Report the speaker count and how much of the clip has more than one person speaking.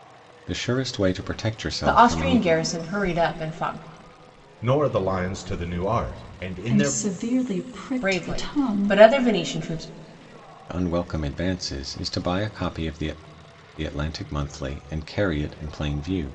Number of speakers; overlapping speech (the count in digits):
4, about 13%